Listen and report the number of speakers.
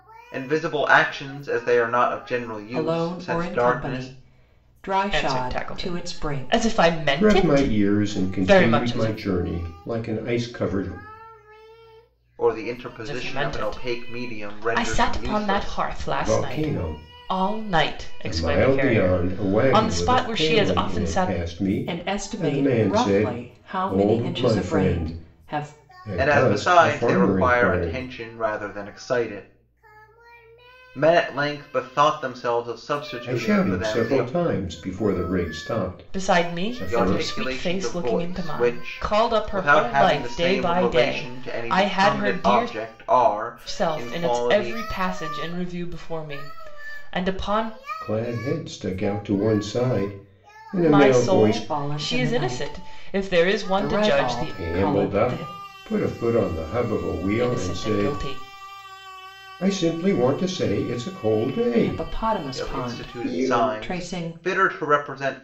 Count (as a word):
four